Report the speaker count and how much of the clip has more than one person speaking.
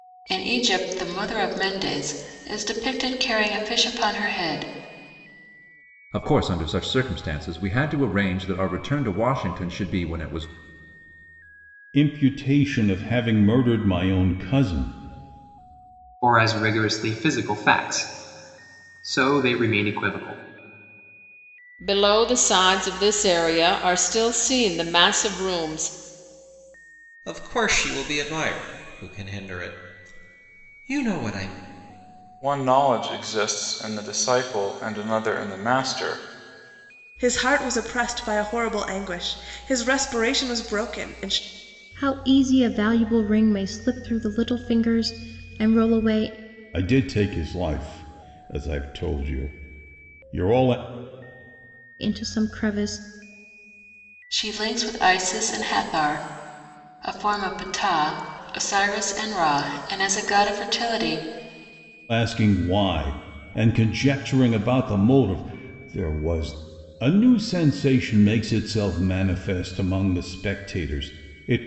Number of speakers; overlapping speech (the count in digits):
9, no overlap